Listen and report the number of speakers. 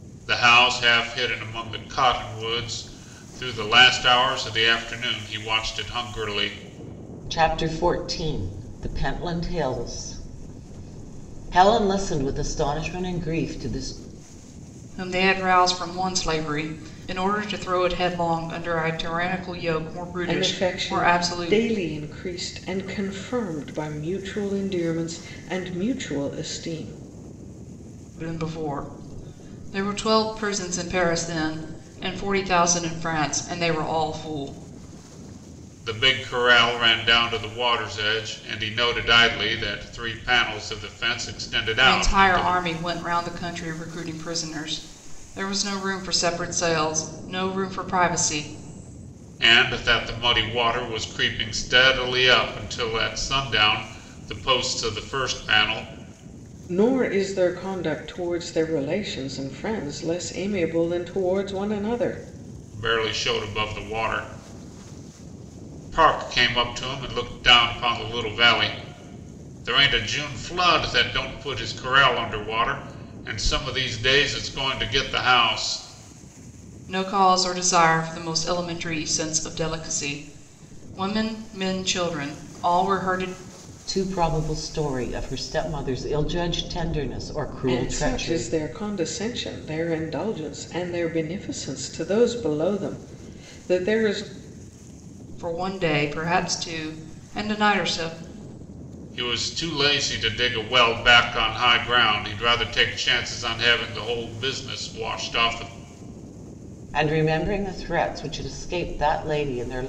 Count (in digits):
4